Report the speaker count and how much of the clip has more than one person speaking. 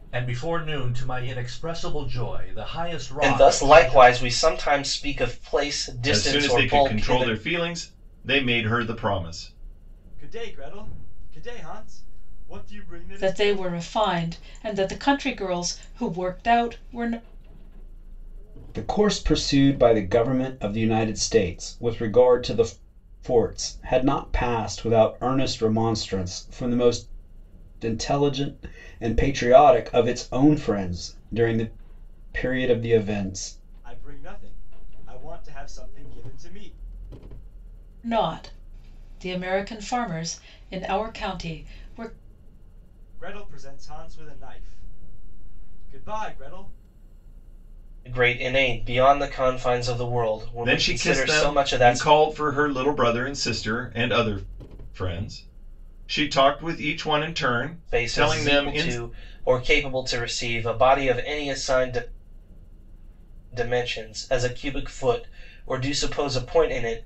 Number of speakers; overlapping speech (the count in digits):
6, about 8%